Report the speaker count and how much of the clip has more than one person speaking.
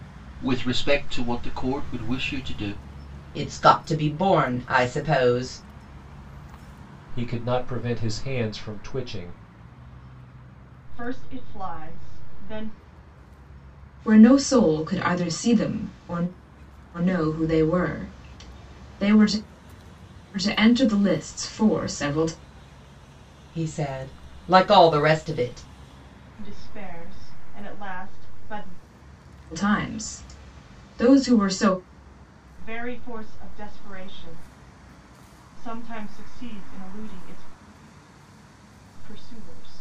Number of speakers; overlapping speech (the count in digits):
5, no overlap